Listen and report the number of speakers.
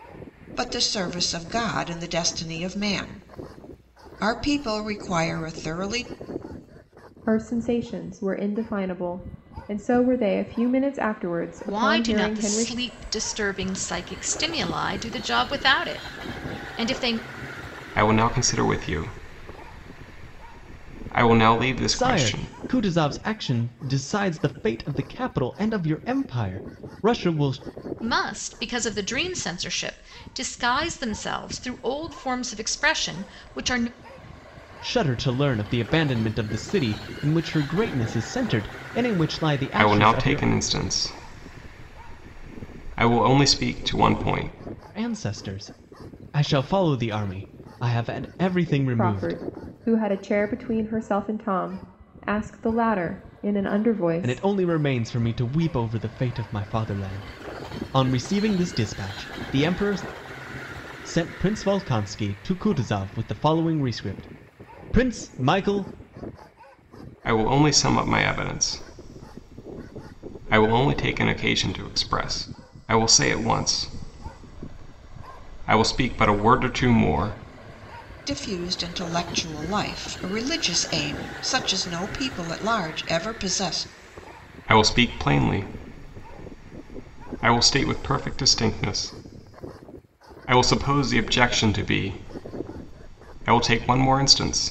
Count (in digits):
5